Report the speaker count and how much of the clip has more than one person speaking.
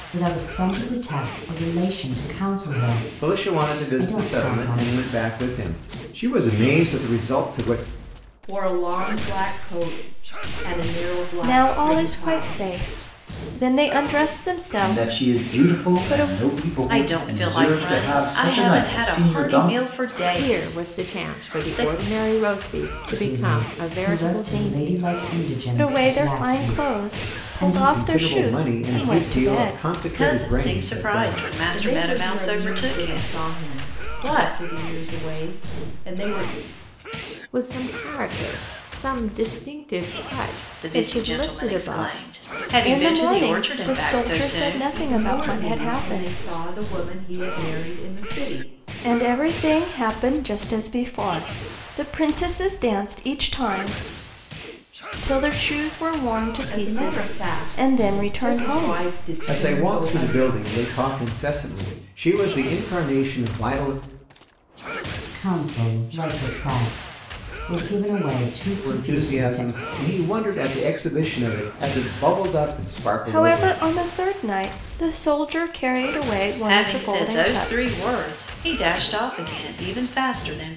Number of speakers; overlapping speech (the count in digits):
7, about 38%